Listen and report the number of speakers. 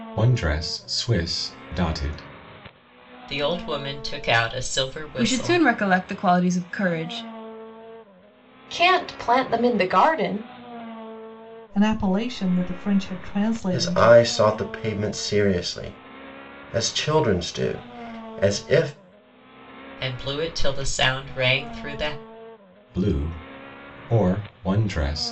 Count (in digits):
6